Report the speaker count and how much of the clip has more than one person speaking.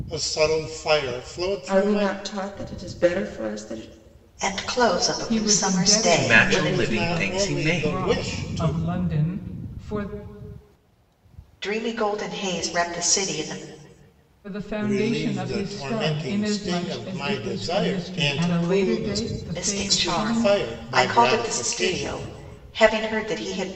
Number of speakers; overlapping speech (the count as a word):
five, about 47%